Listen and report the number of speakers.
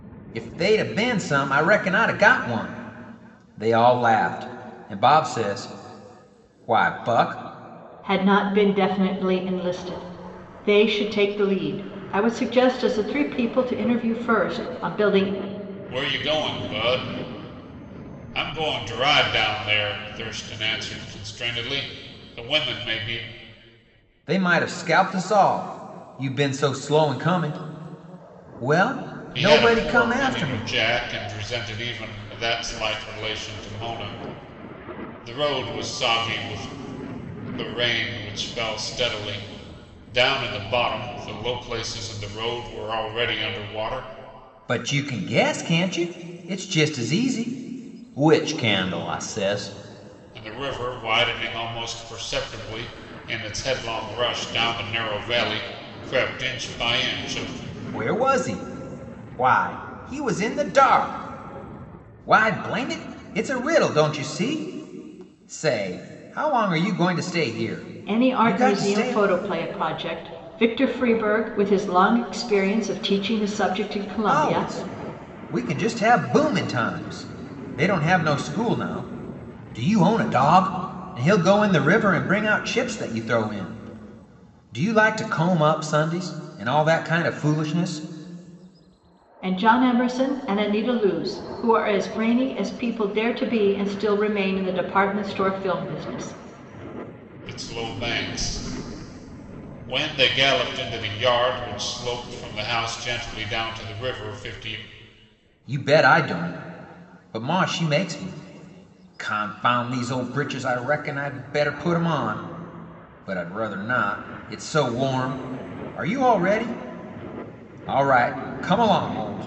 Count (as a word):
three